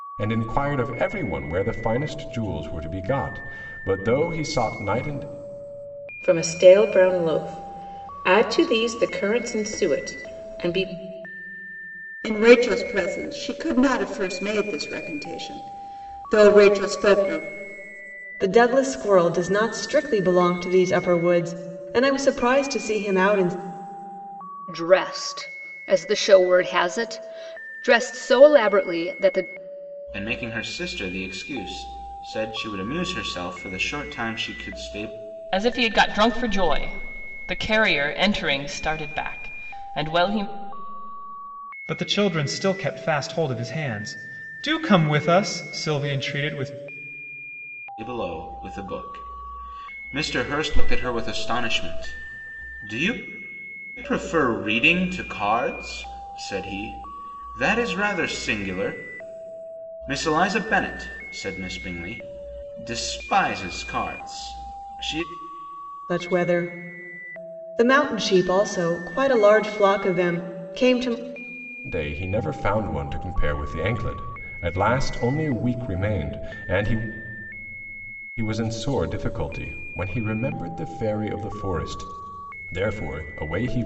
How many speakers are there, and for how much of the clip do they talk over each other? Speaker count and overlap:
8, no overlap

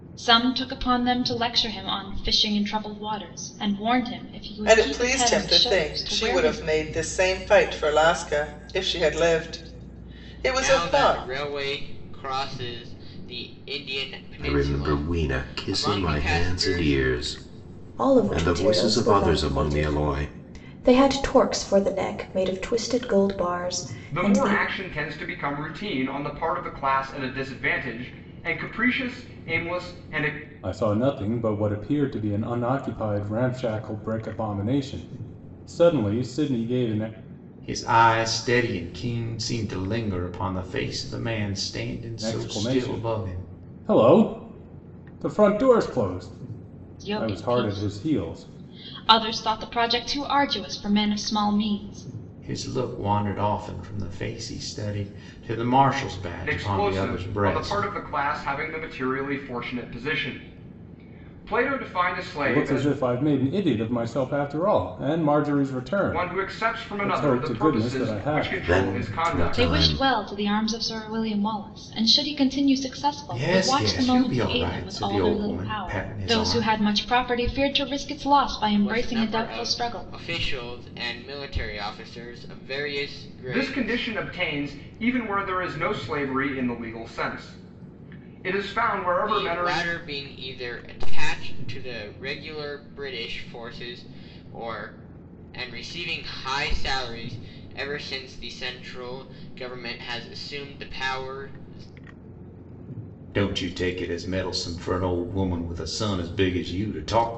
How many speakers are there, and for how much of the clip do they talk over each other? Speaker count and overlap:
8, about 21%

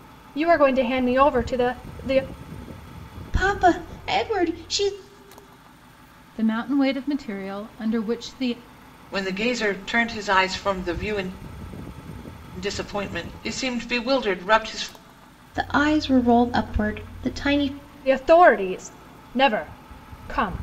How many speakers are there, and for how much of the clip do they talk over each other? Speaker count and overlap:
4, no overlap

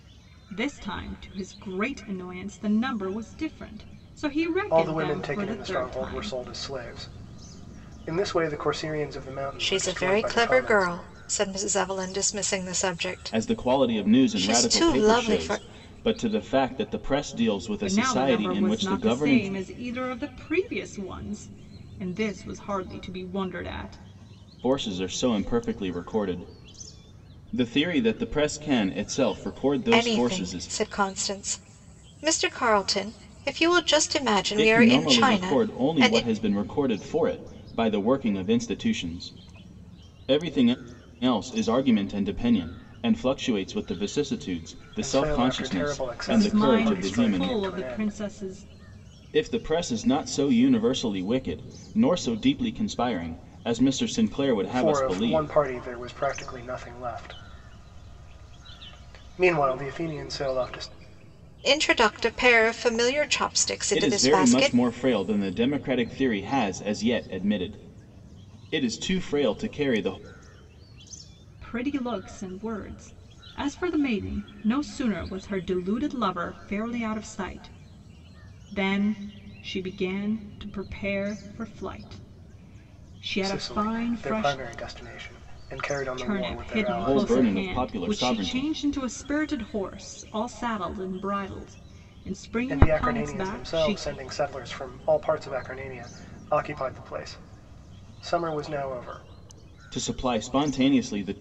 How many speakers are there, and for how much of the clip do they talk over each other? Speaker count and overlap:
4, about 20%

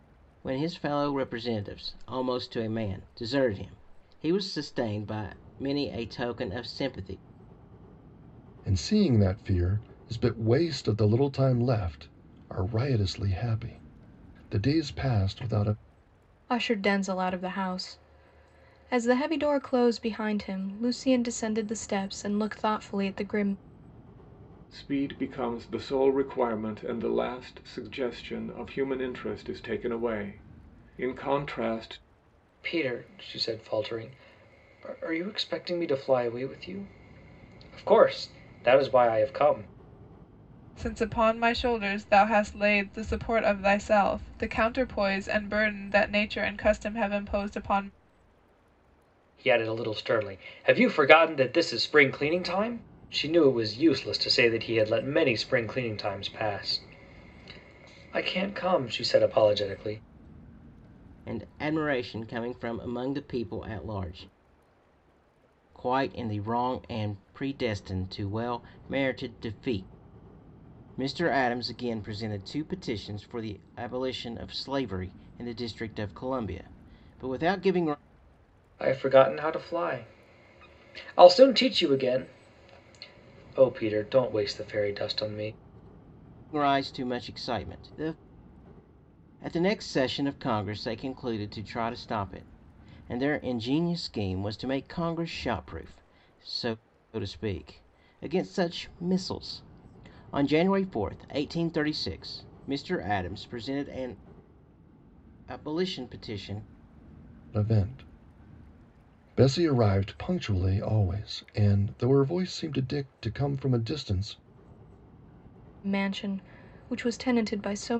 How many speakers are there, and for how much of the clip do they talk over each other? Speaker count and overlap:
6, no overlap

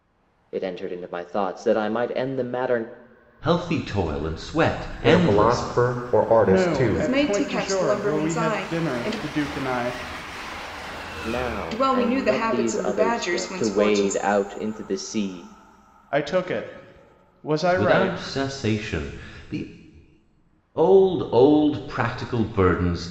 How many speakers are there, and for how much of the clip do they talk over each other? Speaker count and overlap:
5, about 28%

